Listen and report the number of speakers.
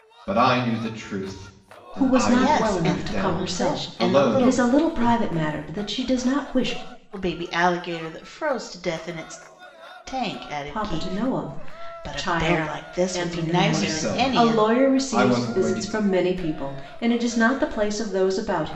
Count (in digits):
3